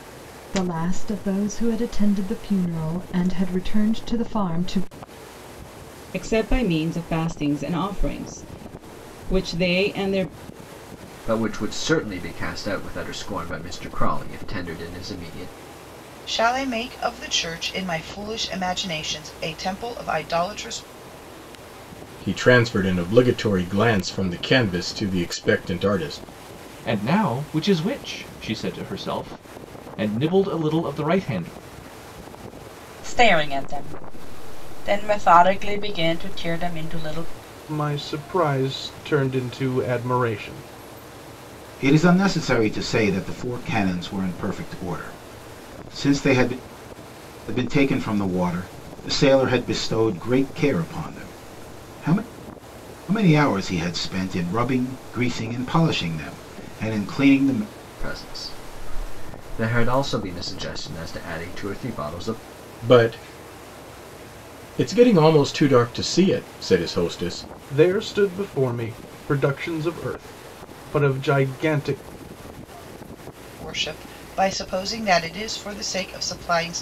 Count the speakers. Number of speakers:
9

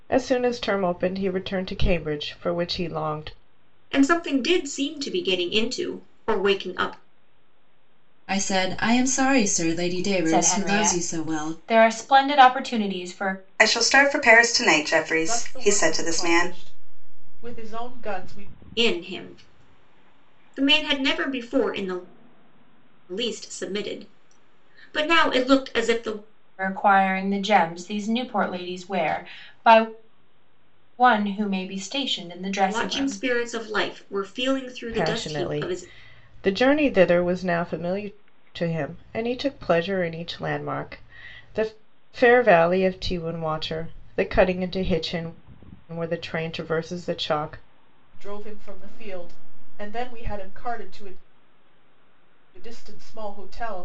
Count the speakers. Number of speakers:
6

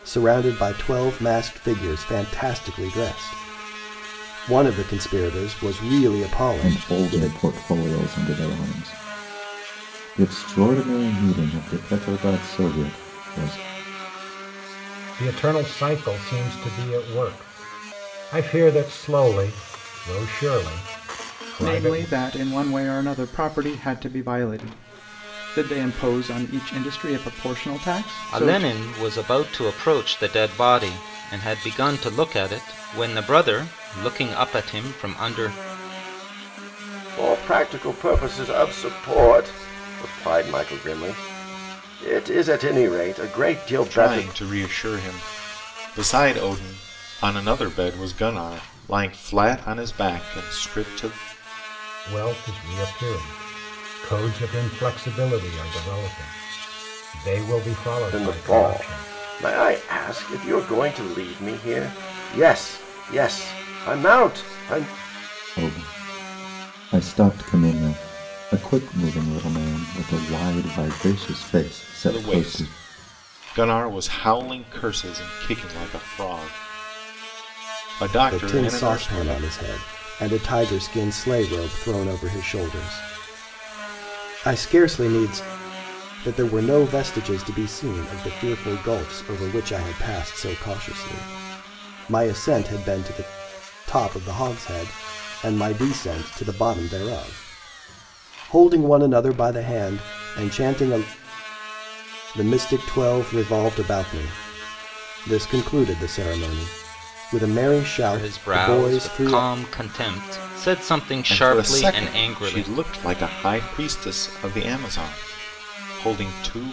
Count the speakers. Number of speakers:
7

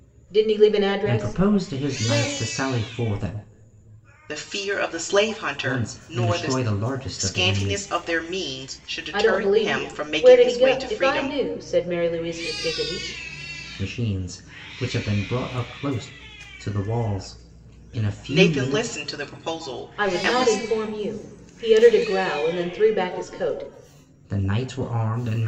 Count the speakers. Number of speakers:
3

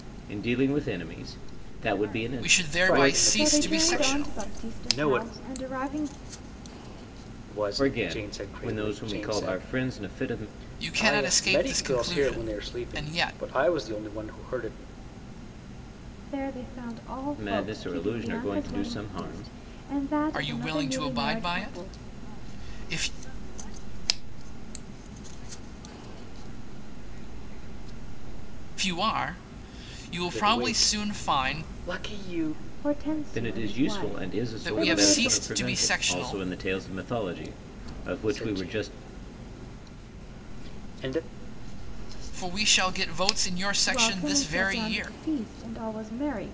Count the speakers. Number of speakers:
5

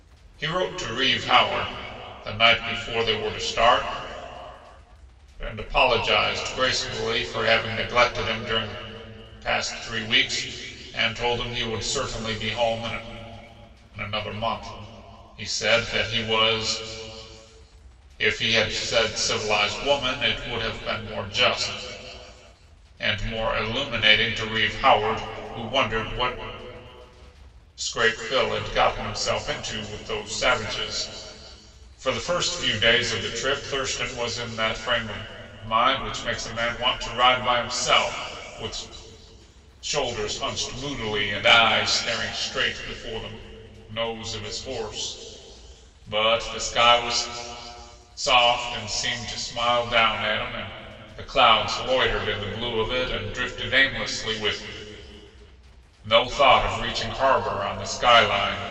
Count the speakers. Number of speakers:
1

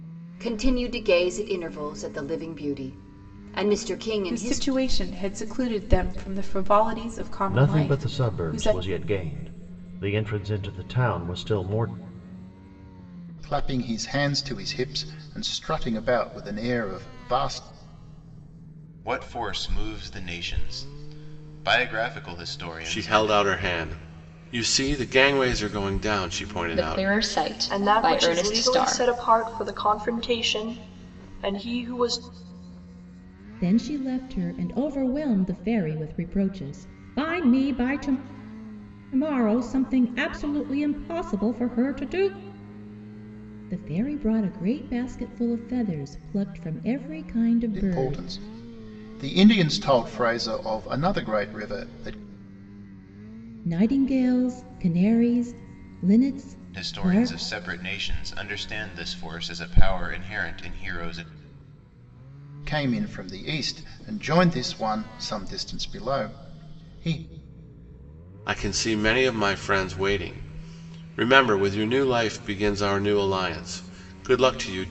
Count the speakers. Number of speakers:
9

